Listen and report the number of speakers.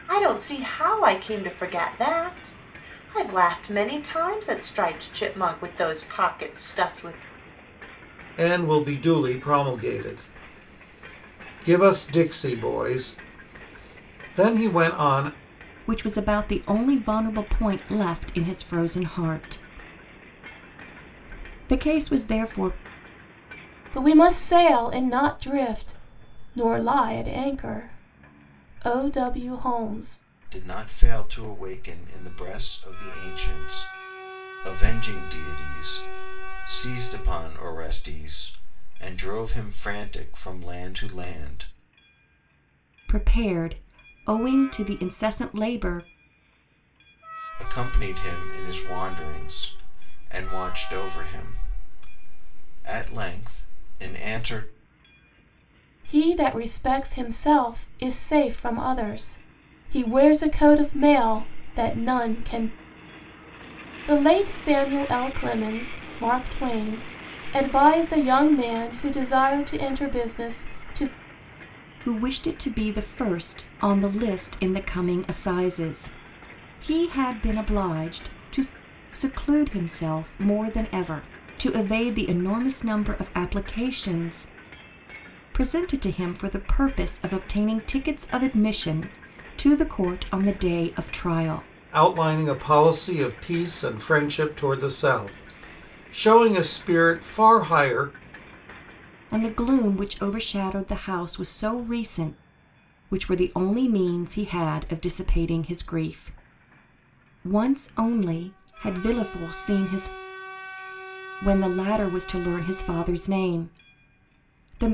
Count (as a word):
five